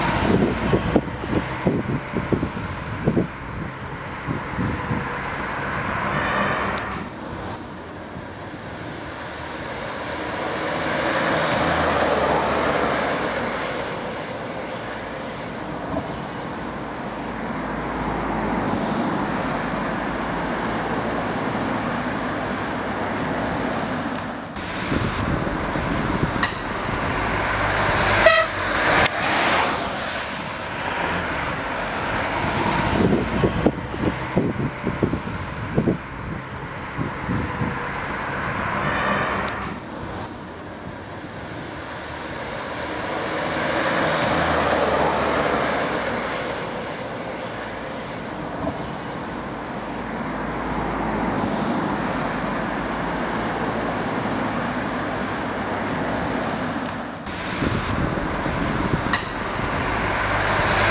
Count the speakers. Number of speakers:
zero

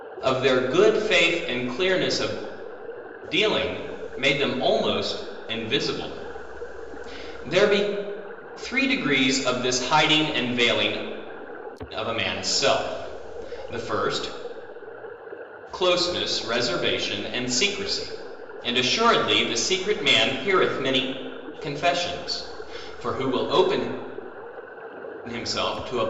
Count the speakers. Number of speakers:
one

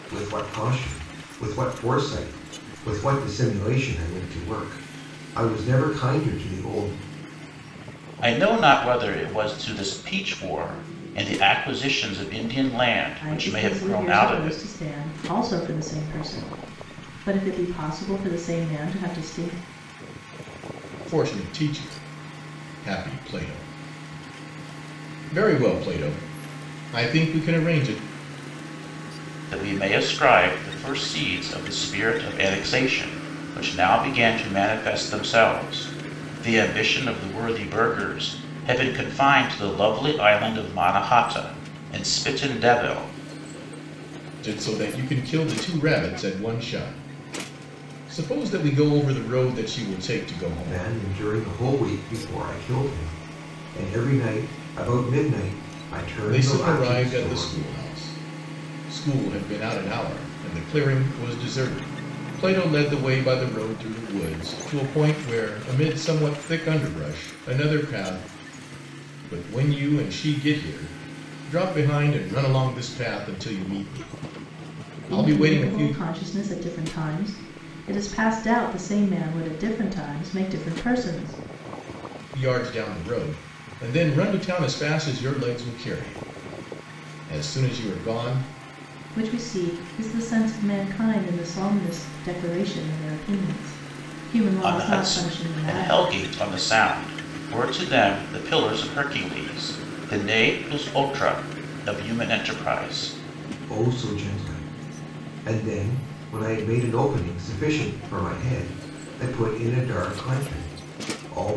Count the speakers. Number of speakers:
four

